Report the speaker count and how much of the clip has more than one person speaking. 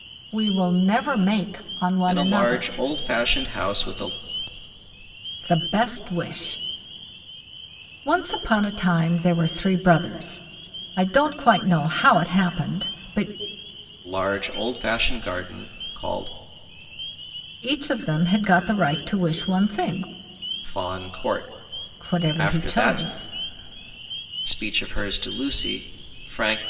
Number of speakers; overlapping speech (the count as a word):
two, about 6%